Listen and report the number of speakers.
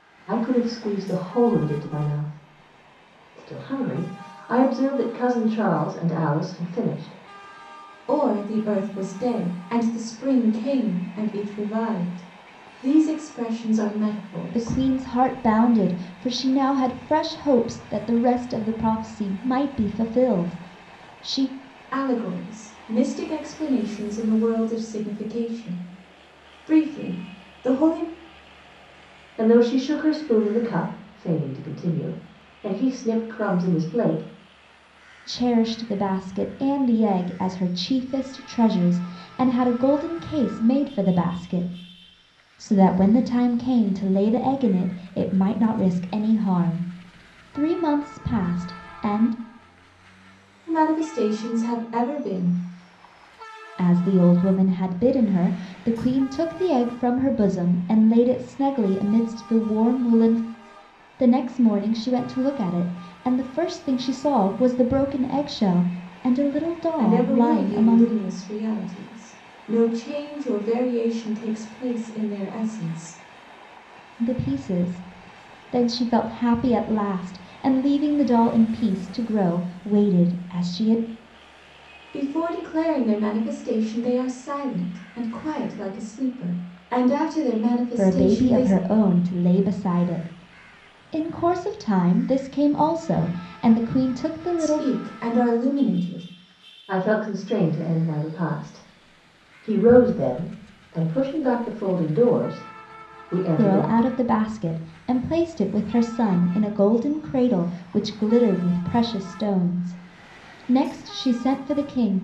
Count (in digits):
3